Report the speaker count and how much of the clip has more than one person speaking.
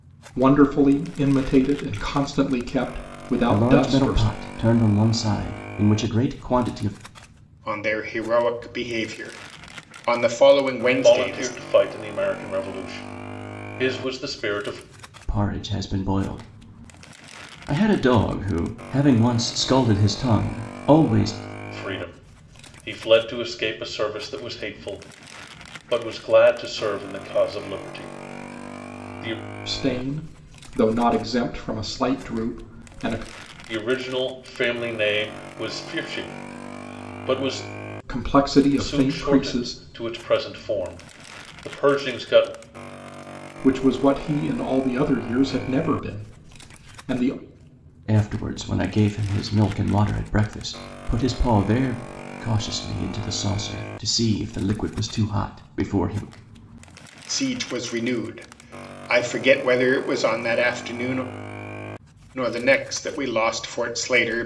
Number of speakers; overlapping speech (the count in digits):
4, about 4%